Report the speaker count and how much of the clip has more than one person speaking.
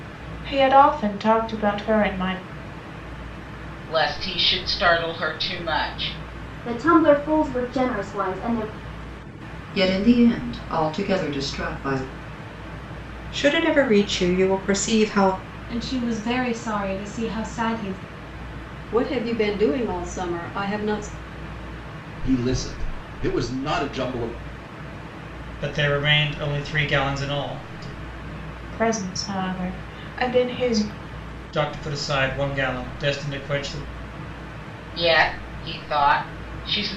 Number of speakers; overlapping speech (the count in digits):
9, no overlap